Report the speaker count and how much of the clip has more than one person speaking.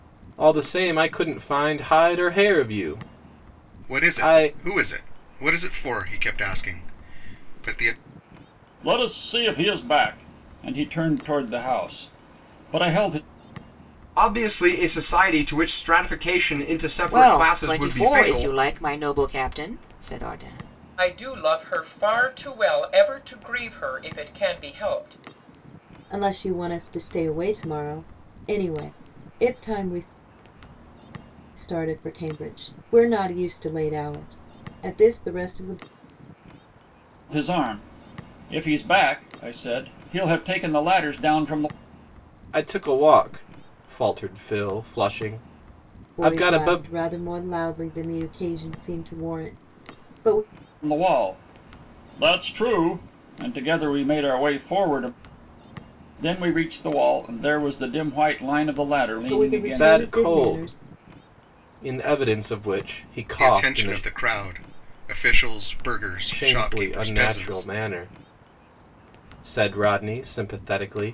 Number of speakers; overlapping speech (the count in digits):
7, about 9%